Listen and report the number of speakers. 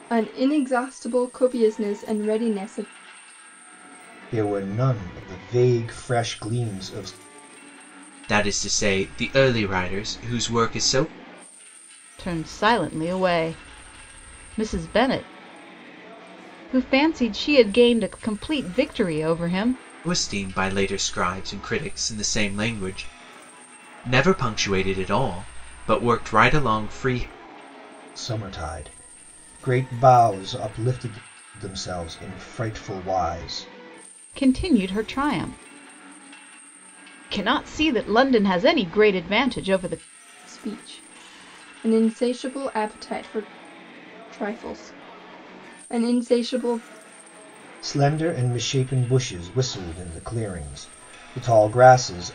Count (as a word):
four